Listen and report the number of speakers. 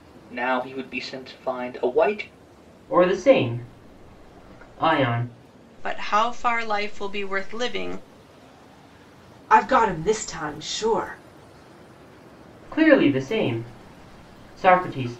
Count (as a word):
four